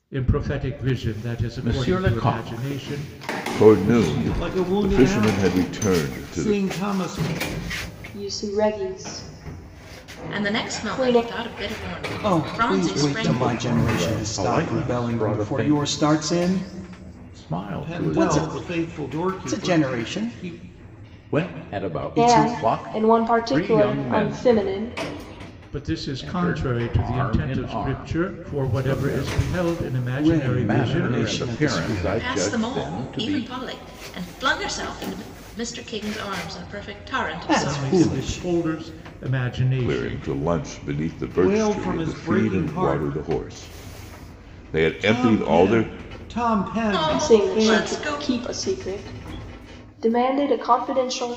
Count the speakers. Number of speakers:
seven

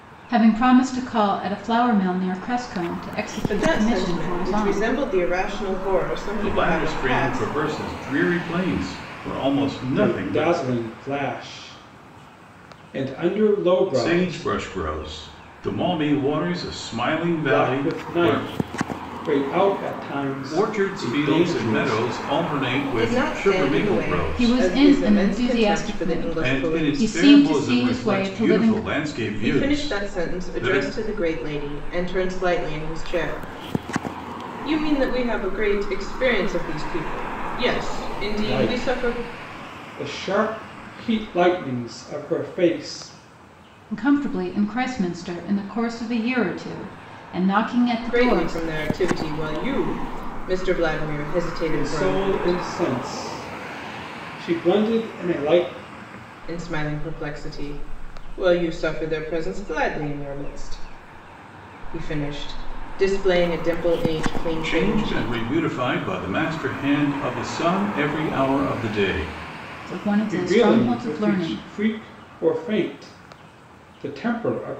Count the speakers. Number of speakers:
four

